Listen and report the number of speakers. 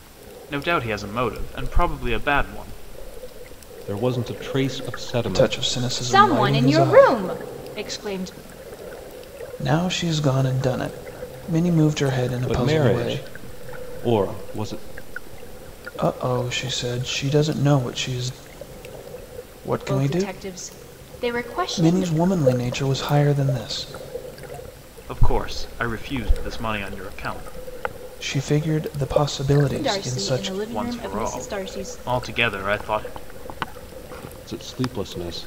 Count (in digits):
4